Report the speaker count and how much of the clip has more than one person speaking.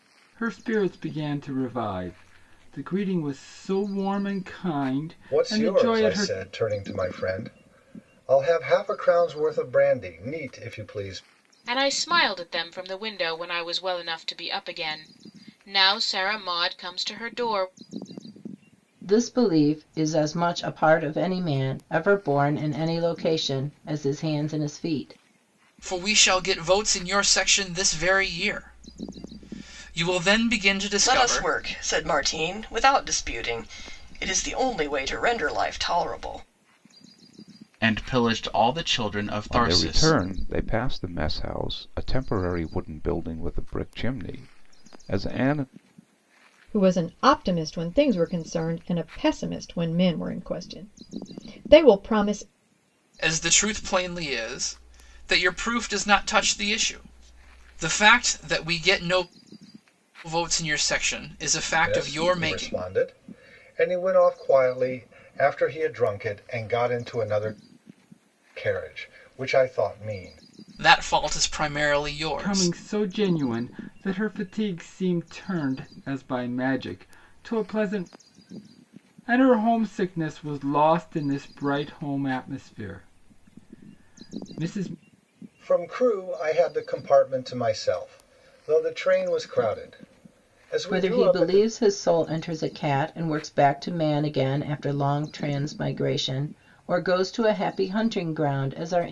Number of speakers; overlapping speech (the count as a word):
nine, about 5%